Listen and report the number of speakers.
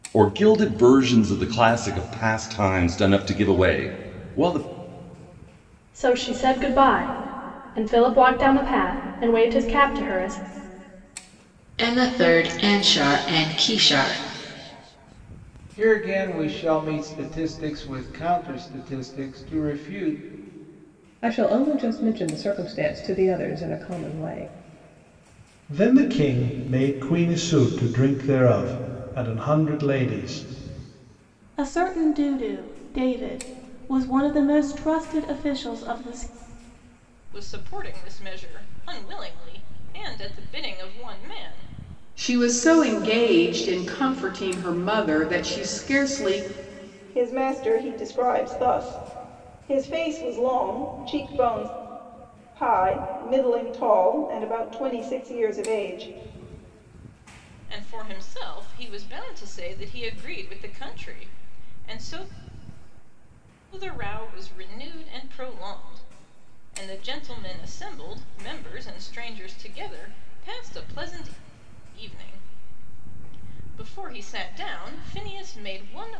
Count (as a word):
ten